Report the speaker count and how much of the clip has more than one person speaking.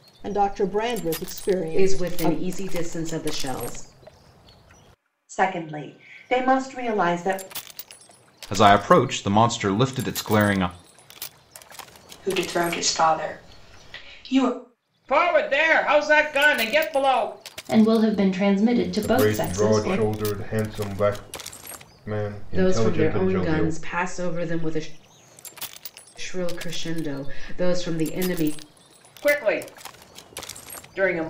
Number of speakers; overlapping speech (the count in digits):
8, about 10%